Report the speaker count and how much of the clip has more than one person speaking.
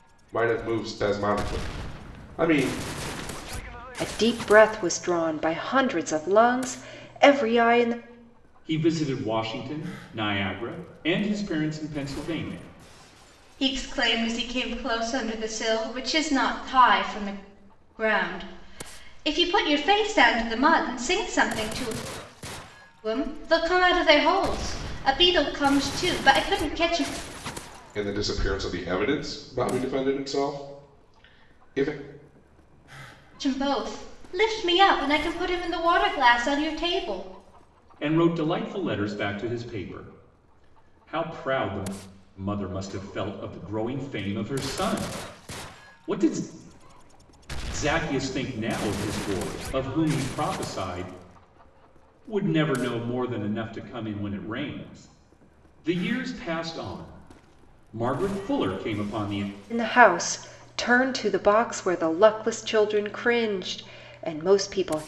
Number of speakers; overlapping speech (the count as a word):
four, no overlap